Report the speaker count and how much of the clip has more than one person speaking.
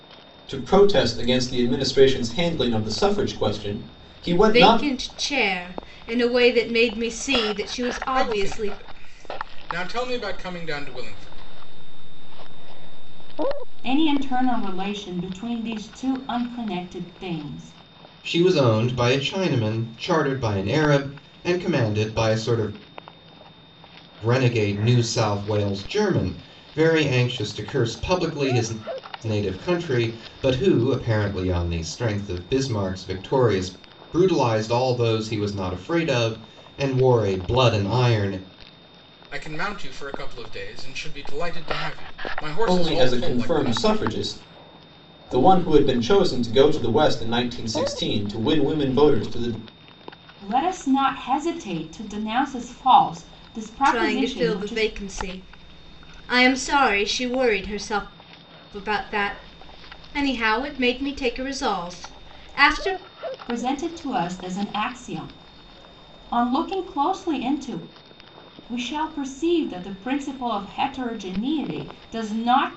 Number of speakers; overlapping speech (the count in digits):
6, about 7%